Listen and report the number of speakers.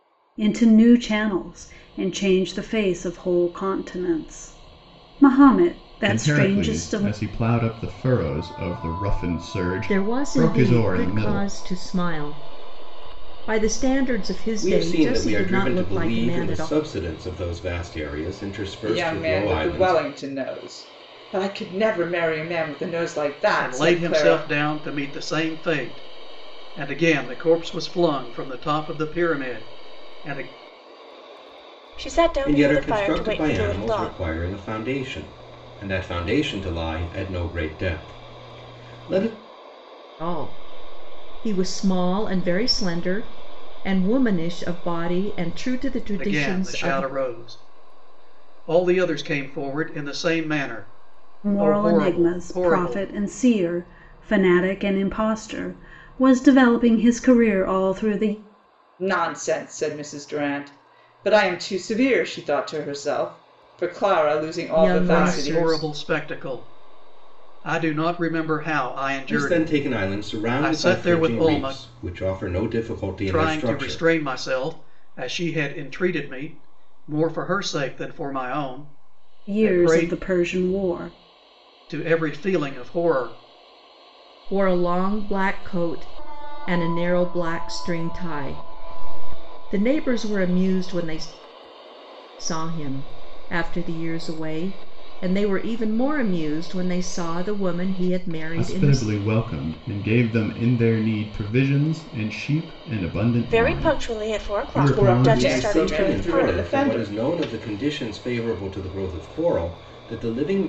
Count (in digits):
7